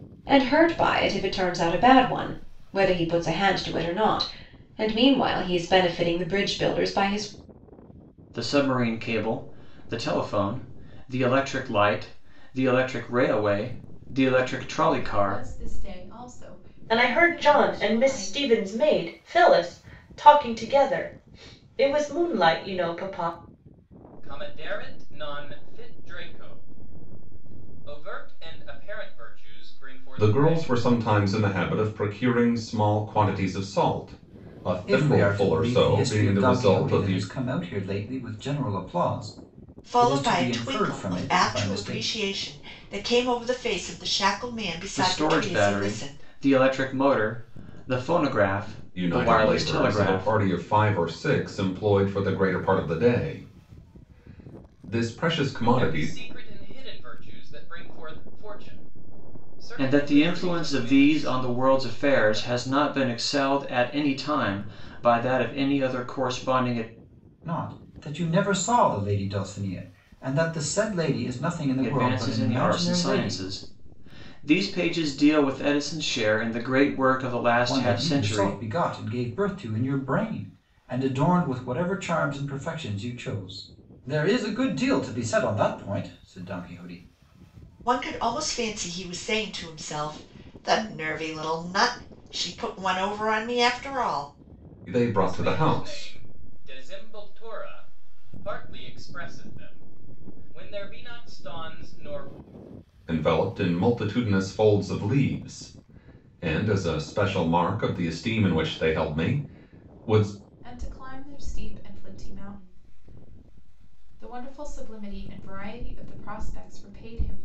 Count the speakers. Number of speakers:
eight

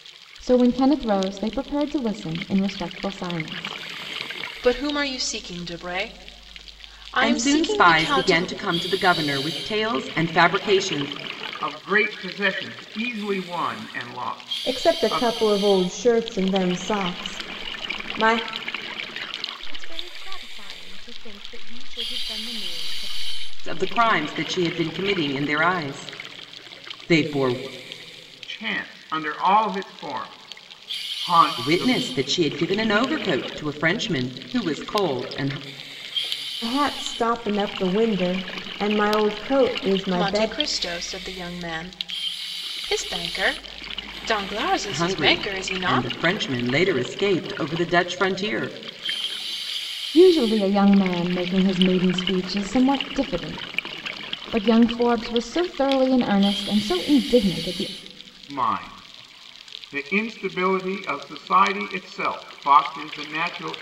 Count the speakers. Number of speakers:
six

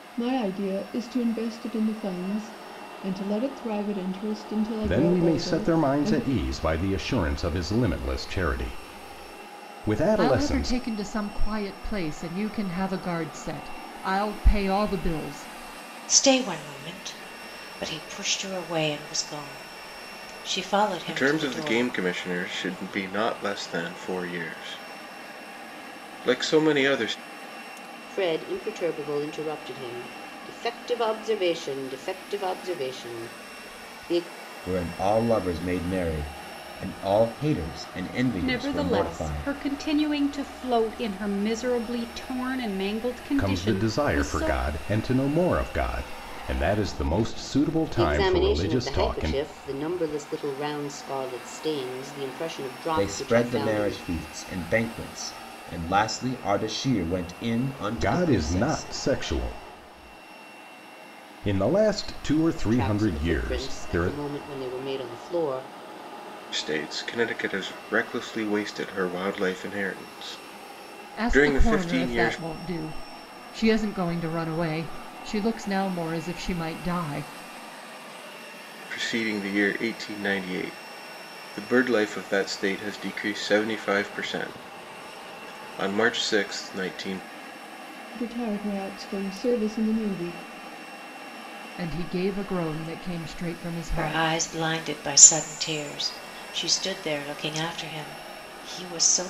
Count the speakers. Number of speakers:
eight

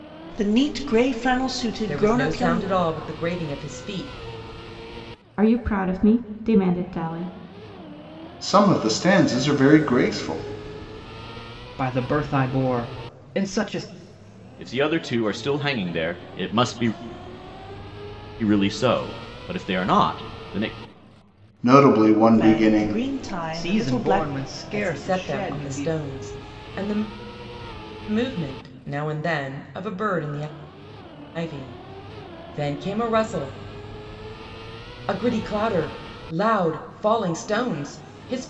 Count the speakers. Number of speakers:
six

